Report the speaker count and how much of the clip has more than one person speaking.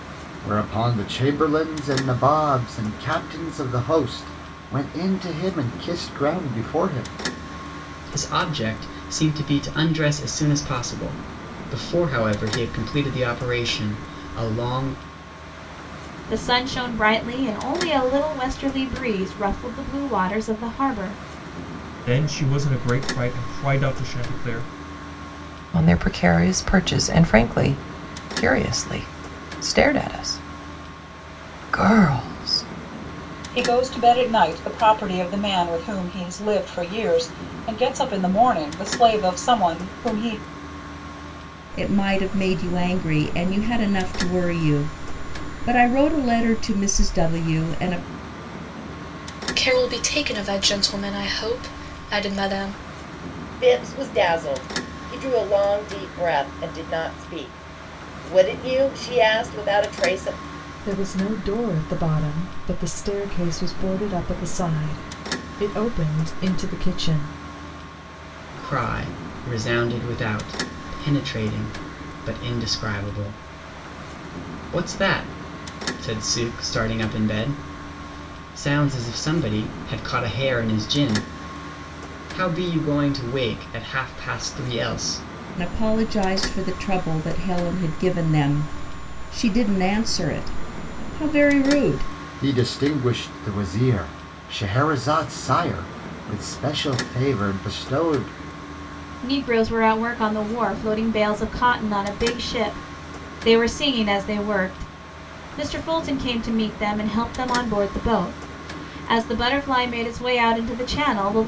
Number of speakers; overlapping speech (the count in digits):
10, no overlap